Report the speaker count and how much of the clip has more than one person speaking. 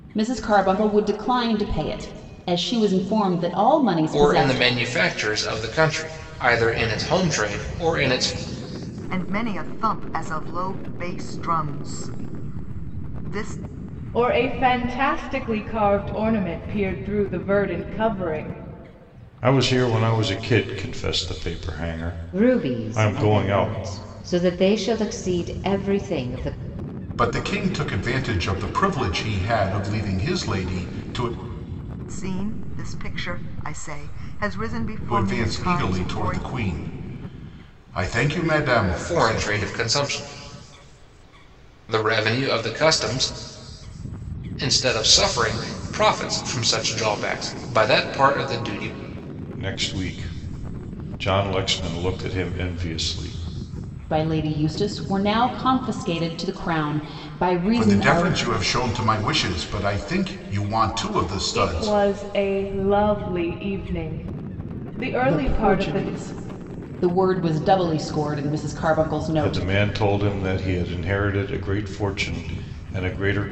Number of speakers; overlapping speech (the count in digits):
7, about 9%